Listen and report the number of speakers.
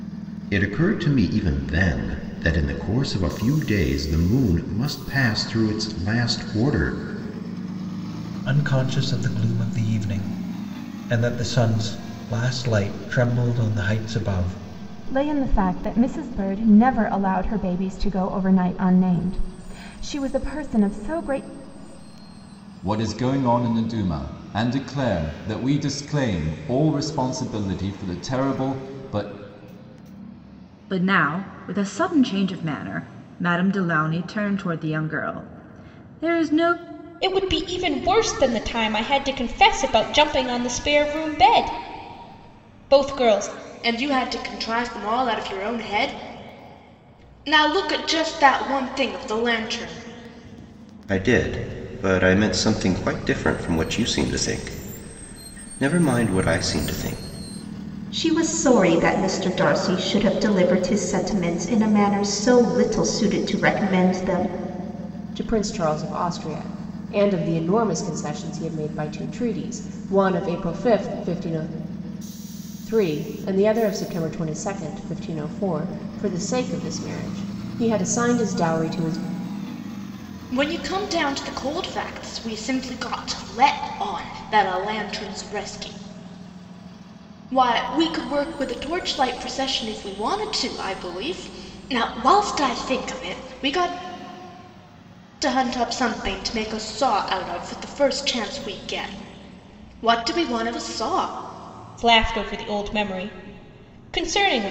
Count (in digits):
10